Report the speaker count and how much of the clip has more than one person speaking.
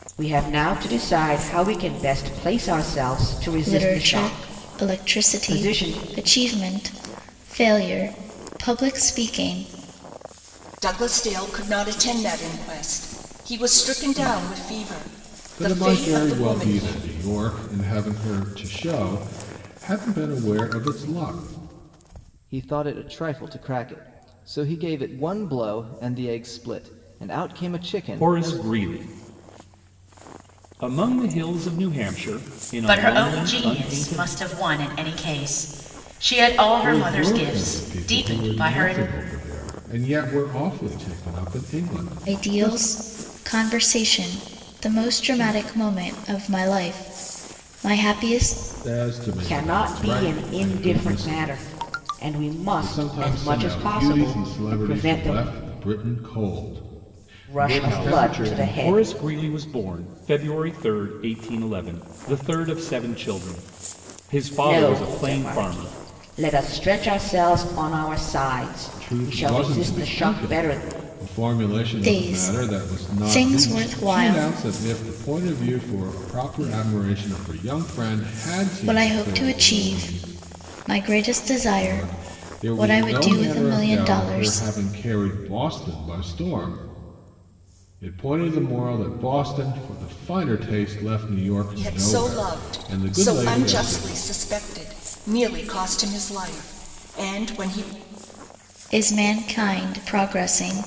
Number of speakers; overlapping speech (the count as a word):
seven, about 27%